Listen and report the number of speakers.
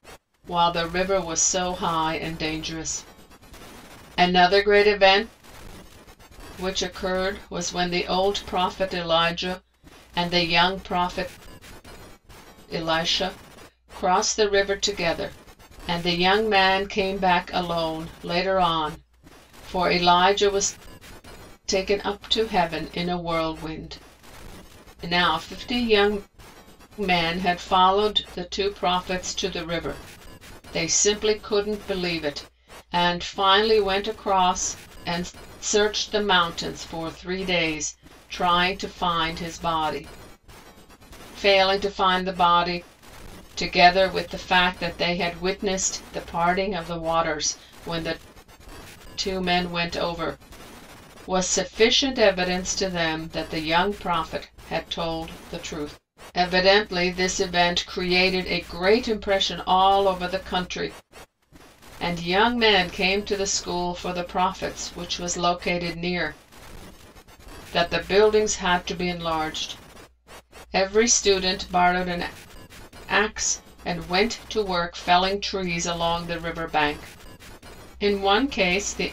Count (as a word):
one